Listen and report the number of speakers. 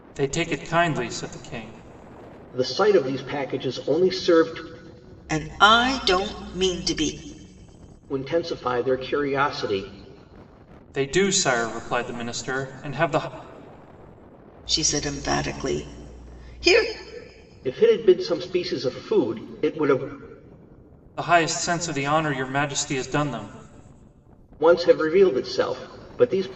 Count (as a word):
three